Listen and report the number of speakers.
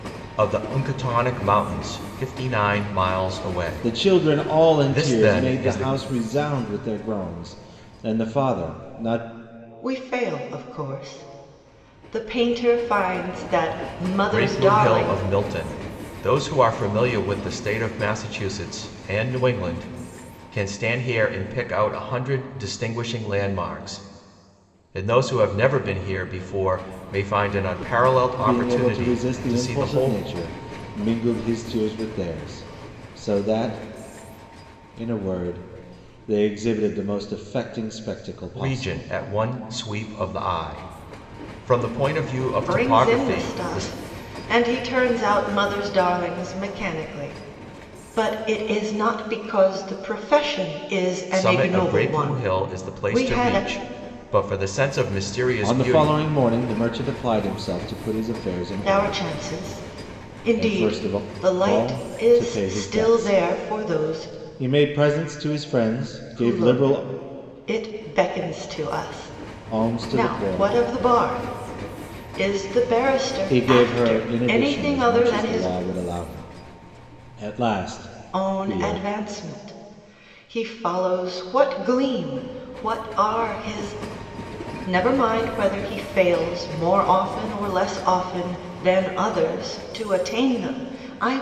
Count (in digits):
3